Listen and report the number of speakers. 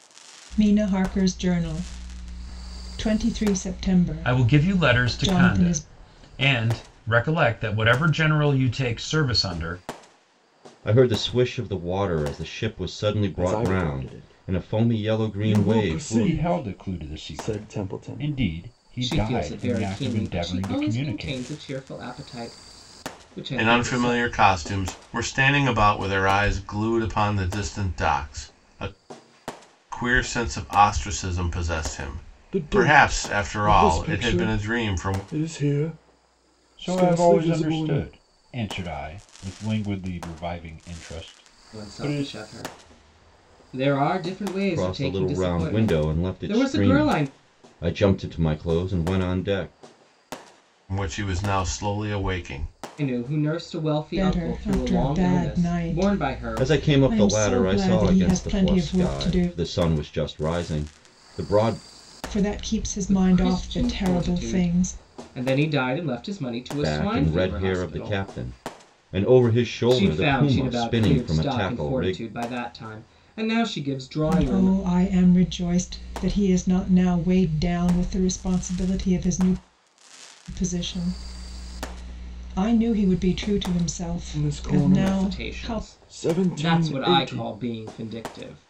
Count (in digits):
7